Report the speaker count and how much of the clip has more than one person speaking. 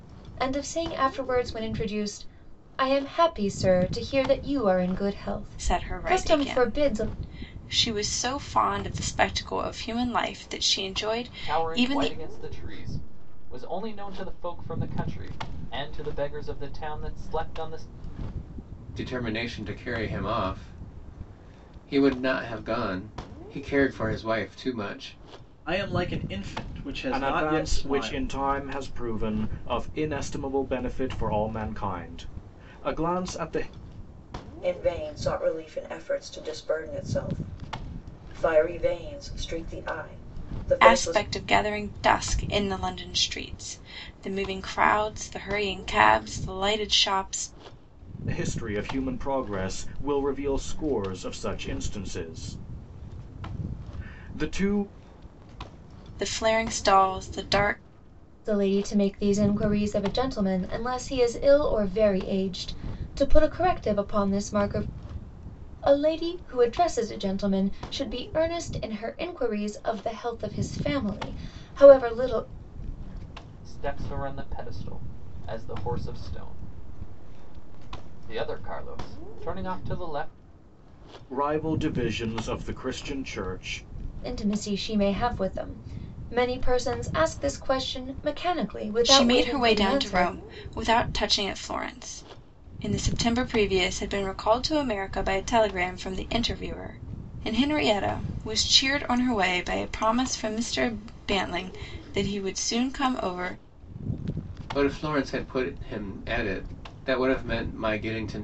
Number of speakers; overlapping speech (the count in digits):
7, about 5%